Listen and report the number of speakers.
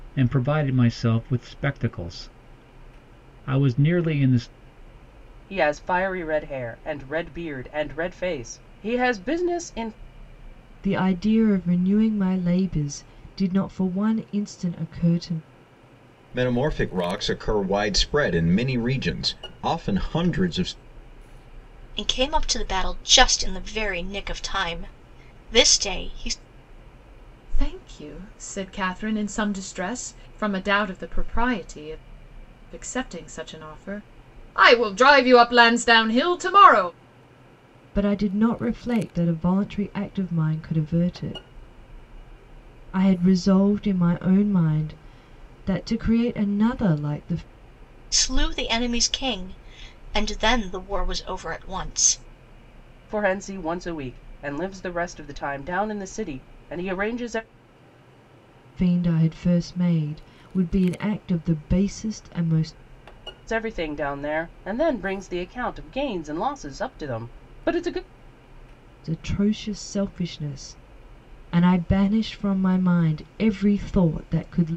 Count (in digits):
6